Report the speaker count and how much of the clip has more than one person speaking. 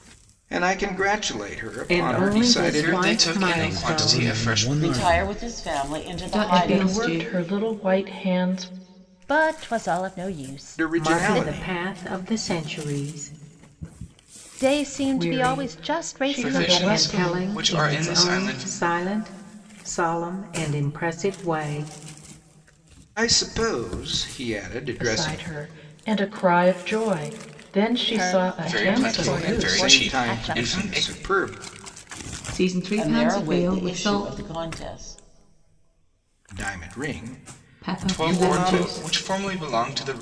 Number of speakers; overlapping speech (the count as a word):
eight, about 38%